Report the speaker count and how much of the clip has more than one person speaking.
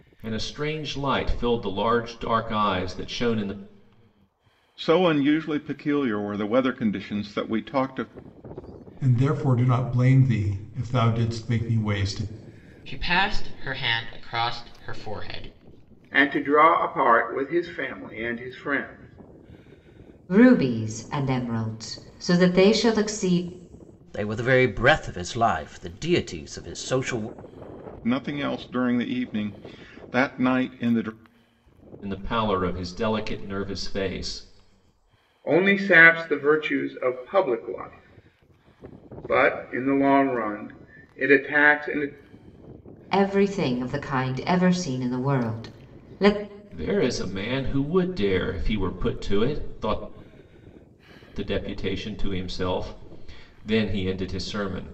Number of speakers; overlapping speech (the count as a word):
seven, no overlap